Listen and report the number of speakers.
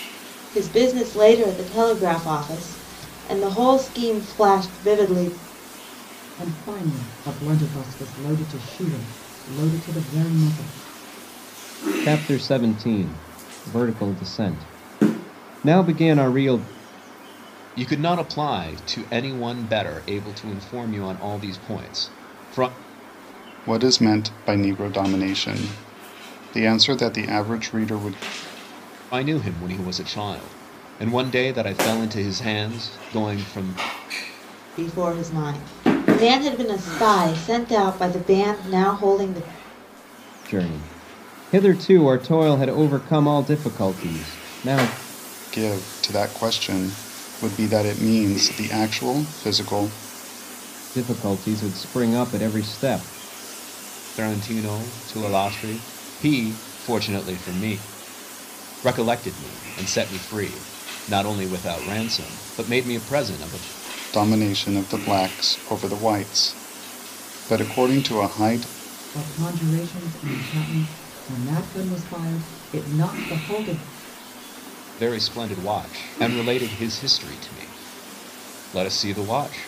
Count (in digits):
5